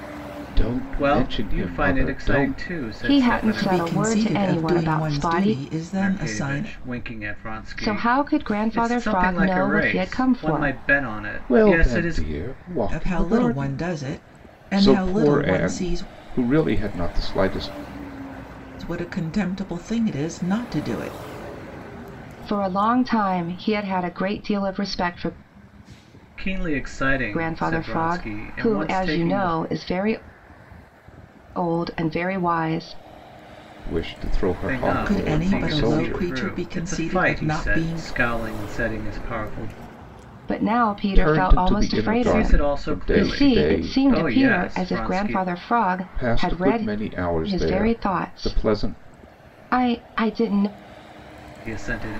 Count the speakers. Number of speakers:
4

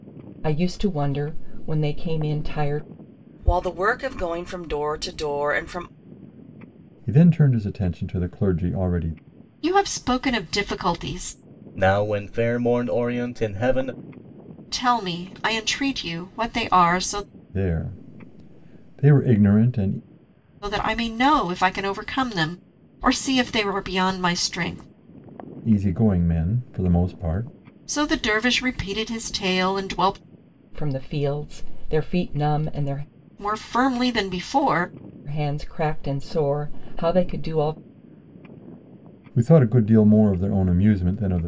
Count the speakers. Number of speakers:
5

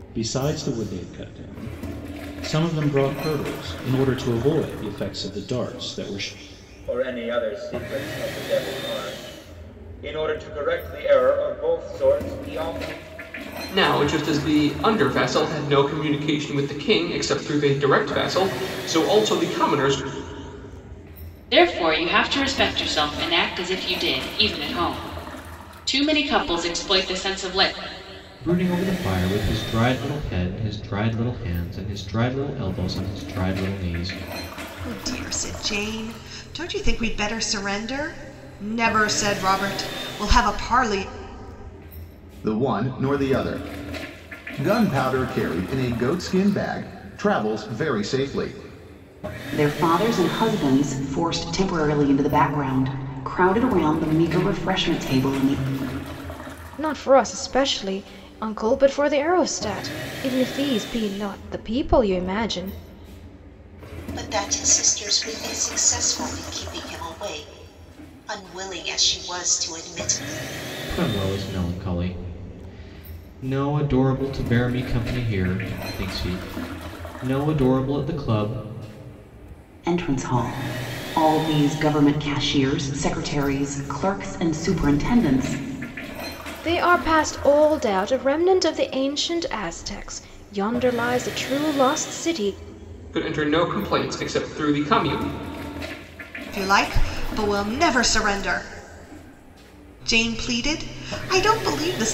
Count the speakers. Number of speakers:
10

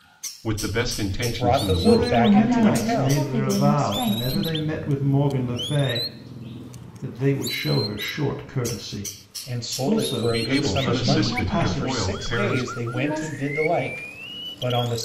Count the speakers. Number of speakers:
4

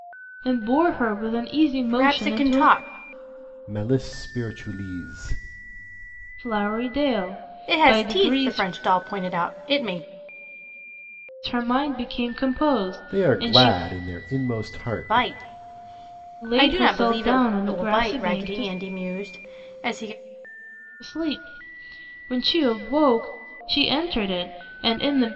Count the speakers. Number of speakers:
3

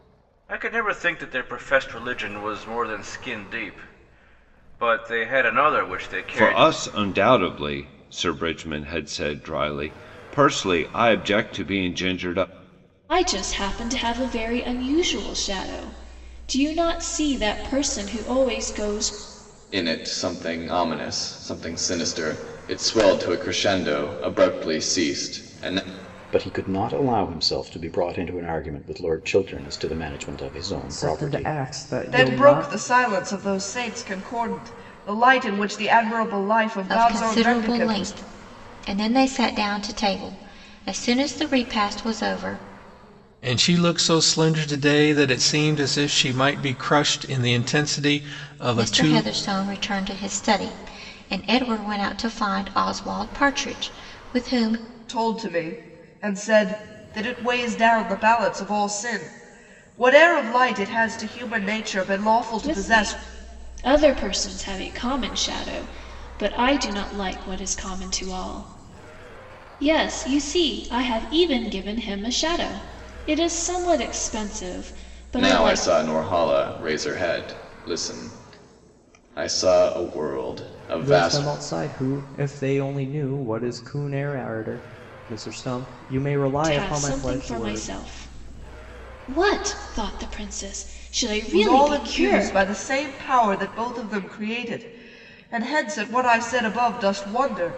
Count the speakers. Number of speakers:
9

